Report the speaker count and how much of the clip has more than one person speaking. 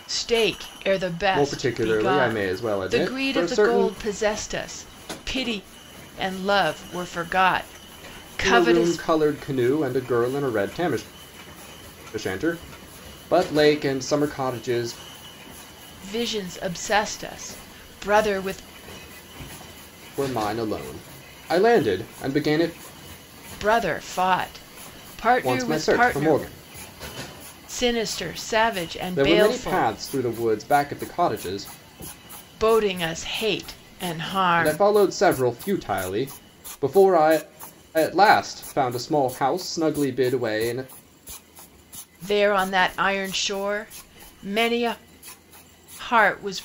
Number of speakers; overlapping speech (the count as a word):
two, about 11%